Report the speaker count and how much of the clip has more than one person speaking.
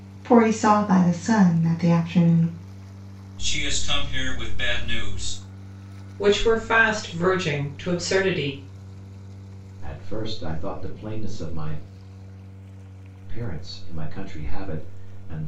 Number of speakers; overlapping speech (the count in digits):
4, no overlap